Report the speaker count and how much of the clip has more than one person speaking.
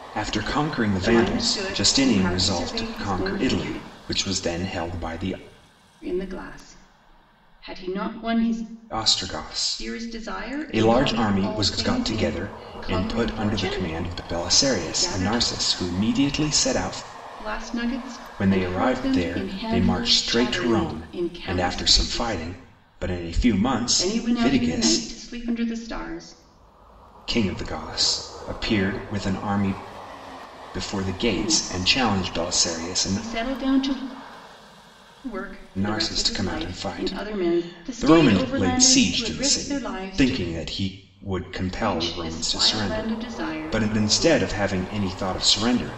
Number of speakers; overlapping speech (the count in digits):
2, about 49%